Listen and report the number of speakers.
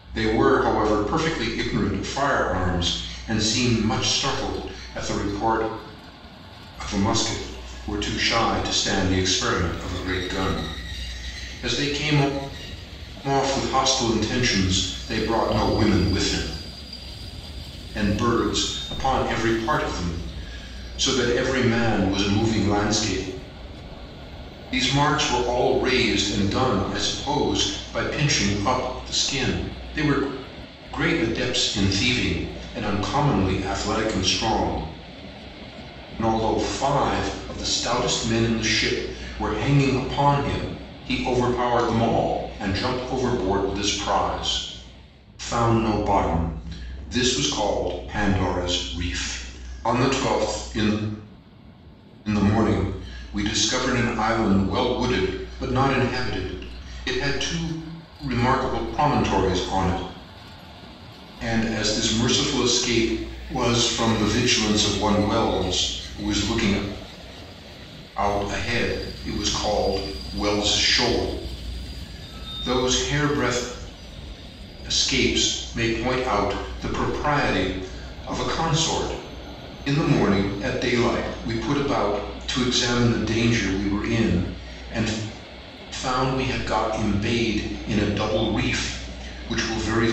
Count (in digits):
1